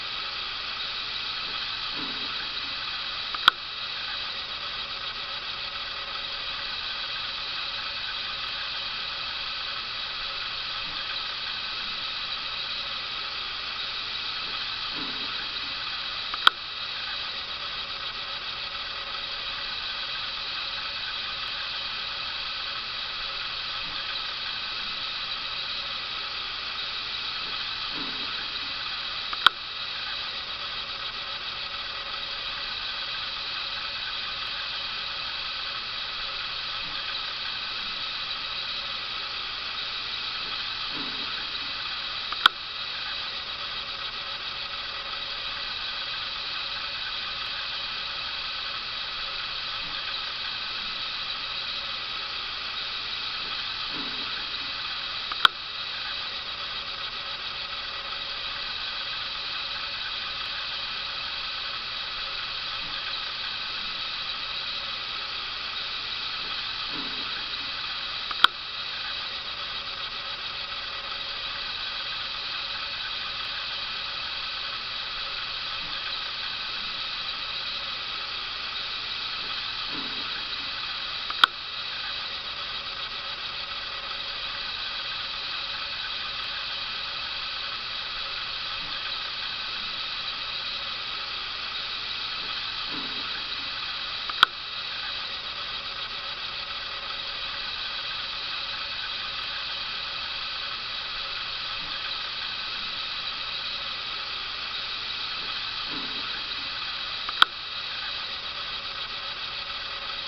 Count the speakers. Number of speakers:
zero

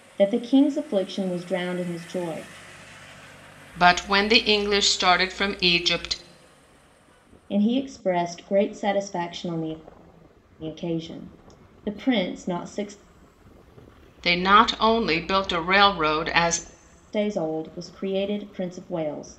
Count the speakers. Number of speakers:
two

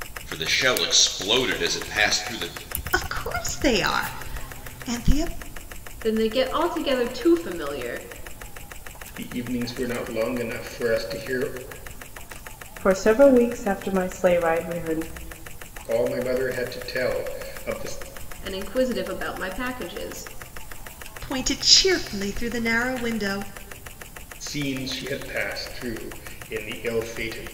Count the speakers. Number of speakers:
five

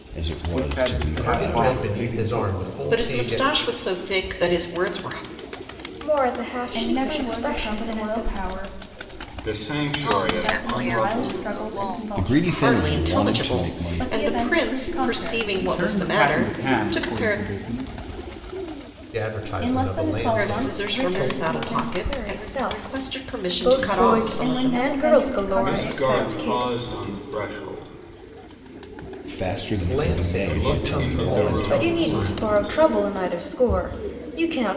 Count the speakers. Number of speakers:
eight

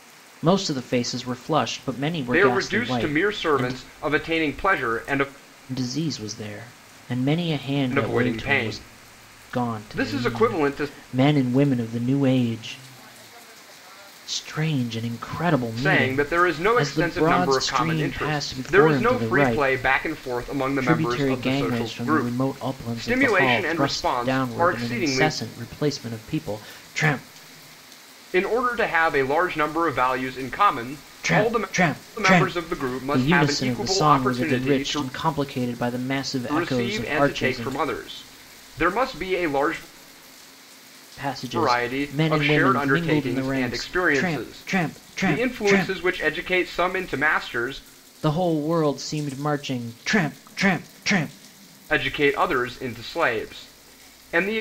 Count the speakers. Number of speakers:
two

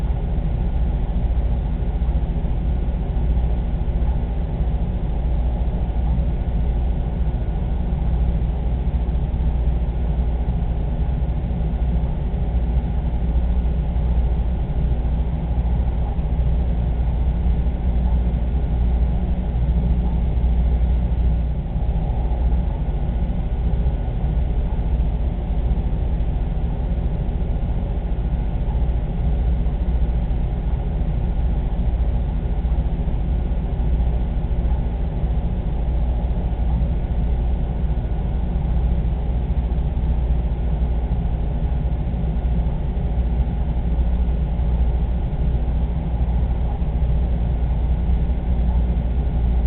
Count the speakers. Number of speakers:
zero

